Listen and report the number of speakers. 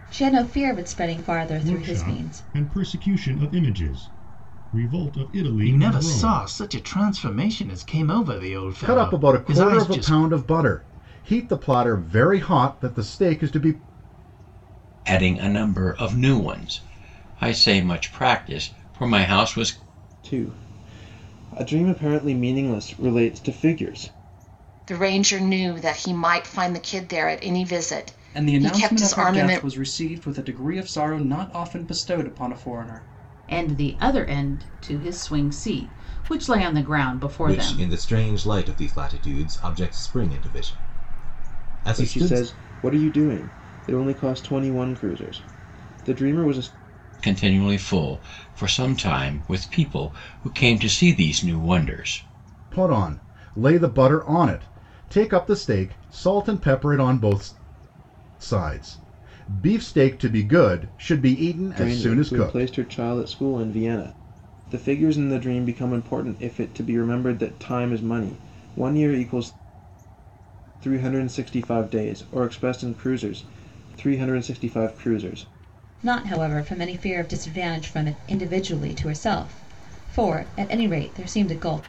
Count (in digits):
10